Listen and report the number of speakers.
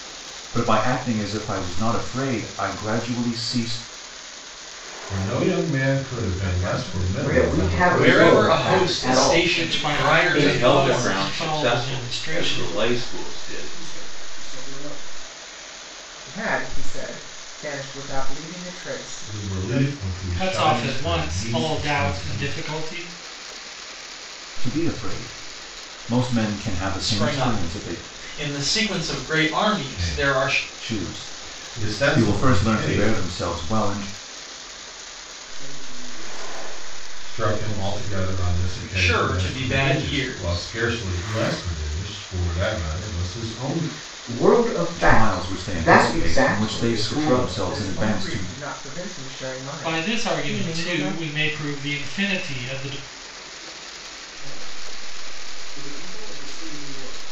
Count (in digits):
8